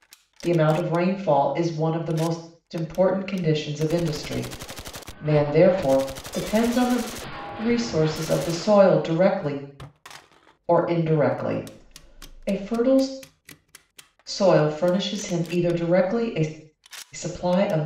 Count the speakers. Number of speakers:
1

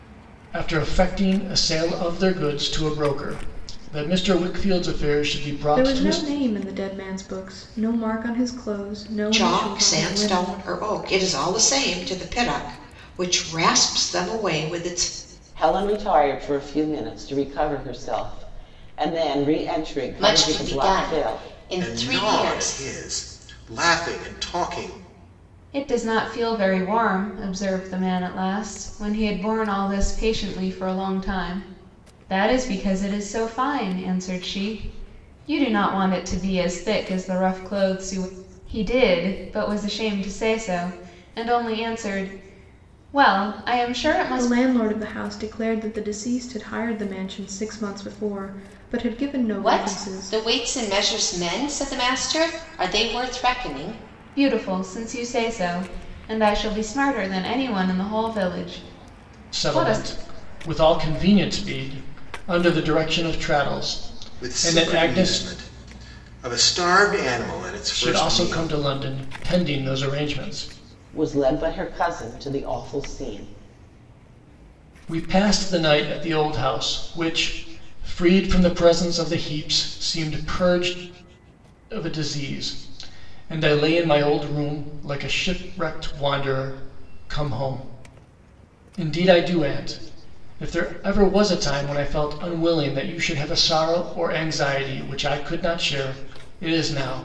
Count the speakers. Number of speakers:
7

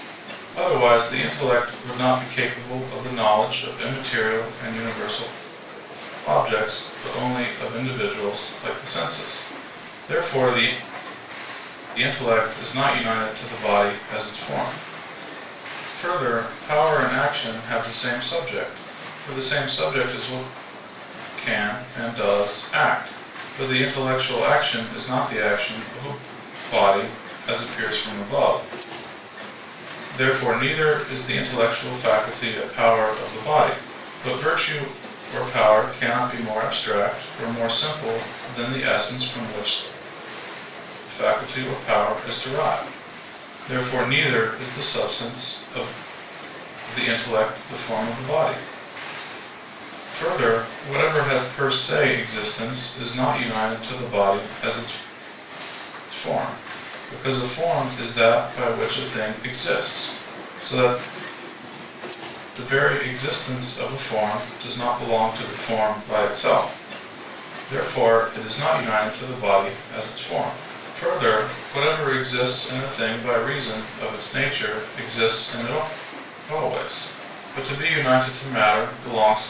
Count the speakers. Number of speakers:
1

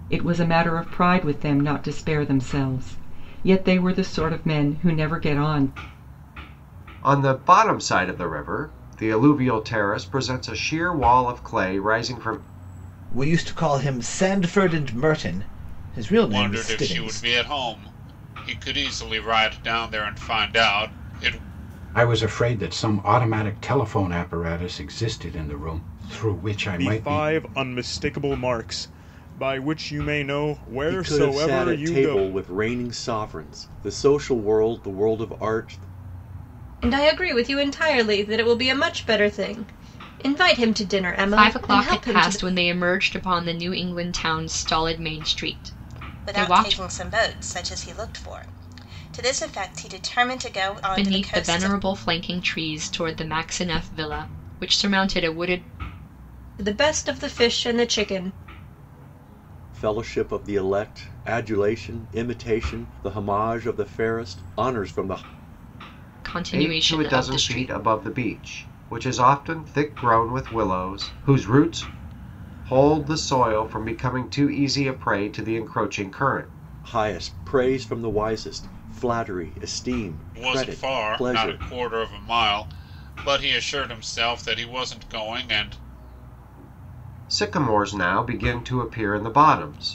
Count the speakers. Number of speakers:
10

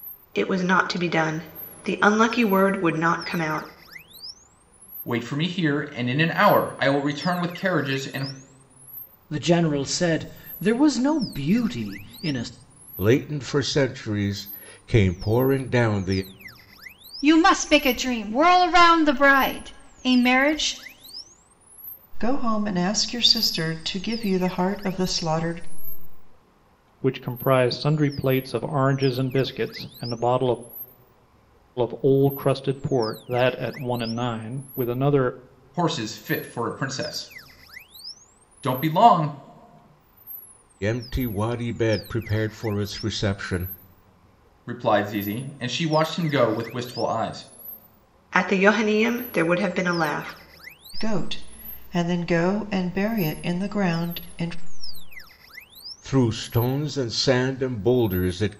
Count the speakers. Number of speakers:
7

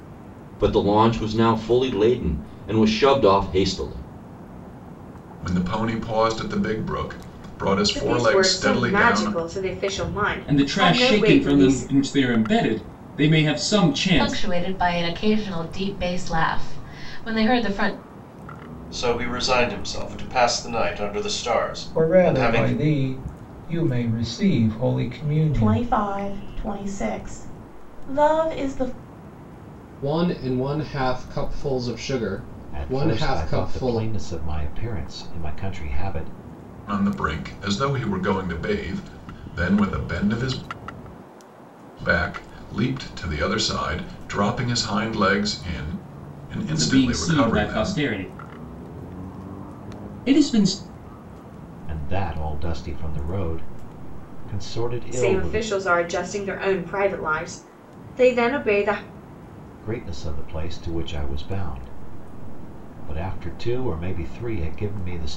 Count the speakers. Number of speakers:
10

